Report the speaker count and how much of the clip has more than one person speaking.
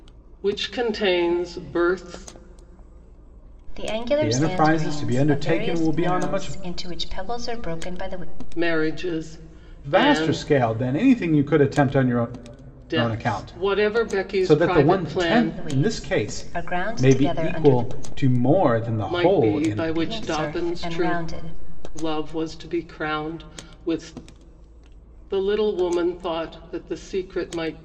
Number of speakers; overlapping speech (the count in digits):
3, about 36%